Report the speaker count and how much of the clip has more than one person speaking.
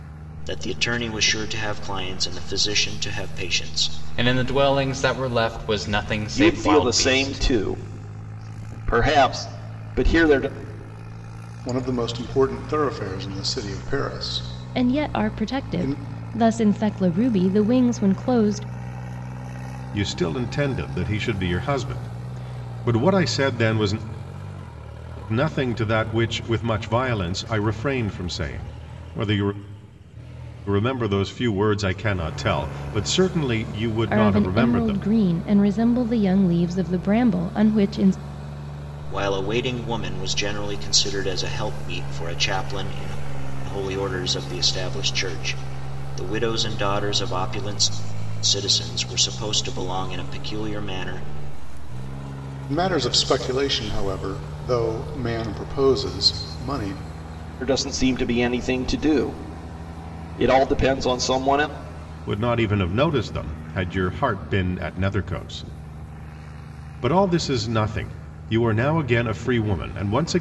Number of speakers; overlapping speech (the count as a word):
six, about 5%